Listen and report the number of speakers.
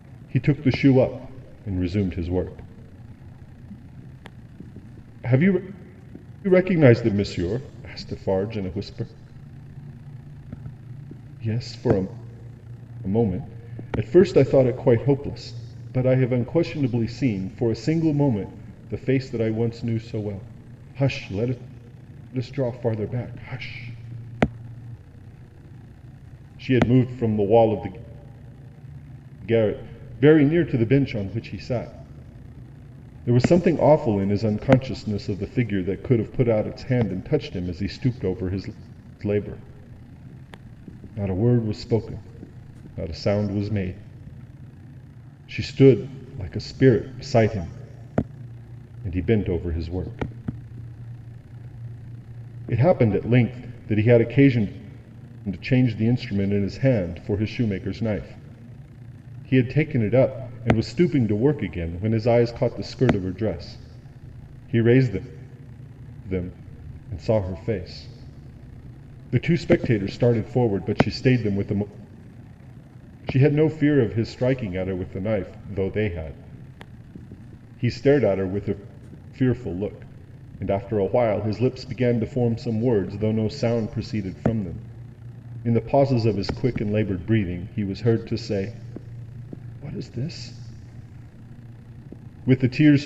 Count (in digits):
1